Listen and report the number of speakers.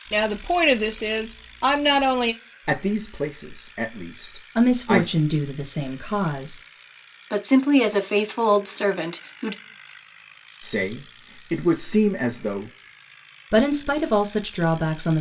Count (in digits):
4